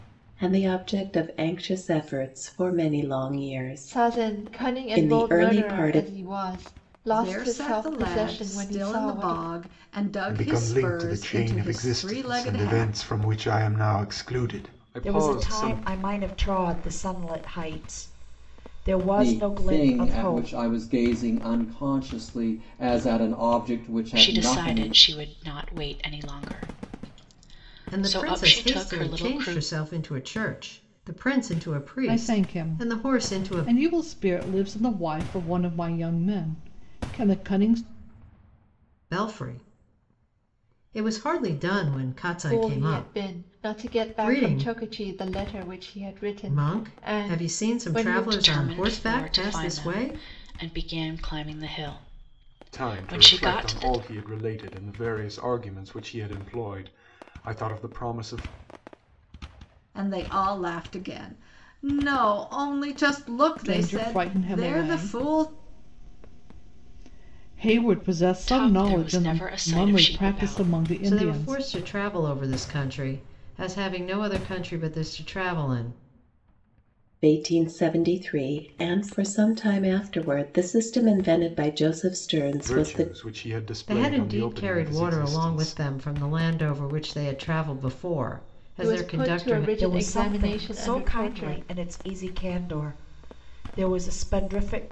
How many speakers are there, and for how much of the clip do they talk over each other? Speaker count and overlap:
nine, about 33%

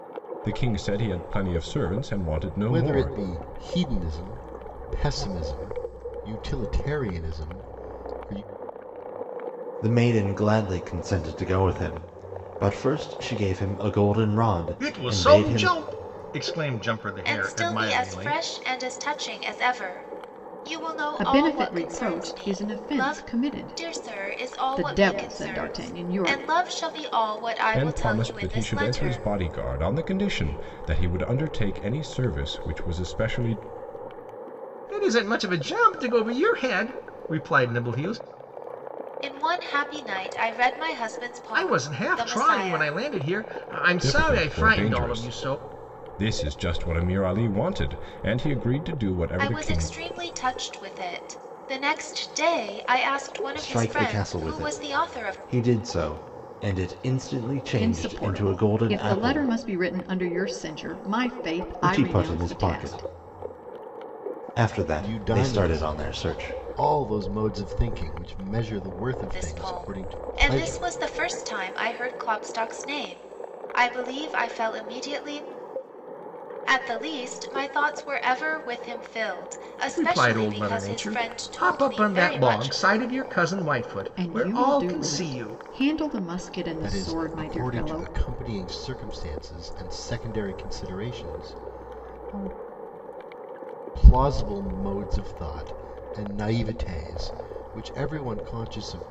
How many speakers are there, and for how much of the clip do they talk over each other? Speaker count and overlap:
six, about 27%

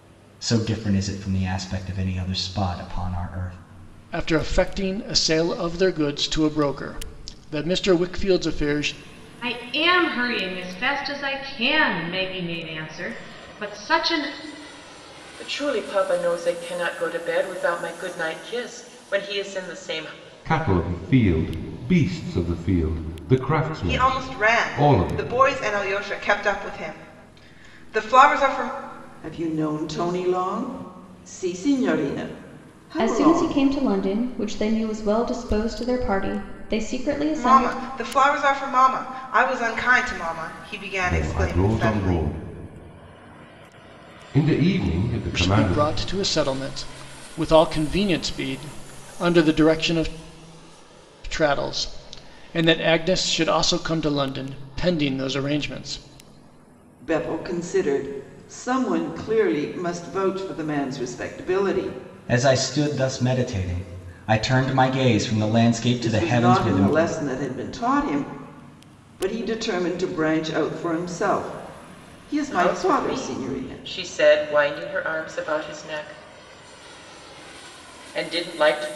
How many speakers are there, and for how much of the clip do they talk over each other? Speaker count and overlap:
eight, about 8%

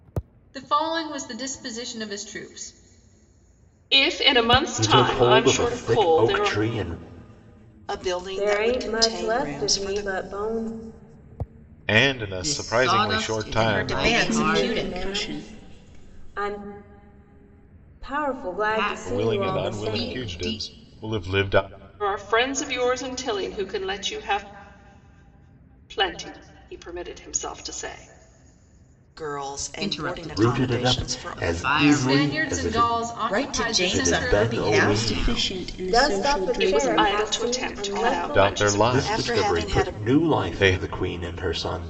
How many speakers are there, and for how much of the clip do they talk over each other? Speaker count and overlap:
nine, about 46%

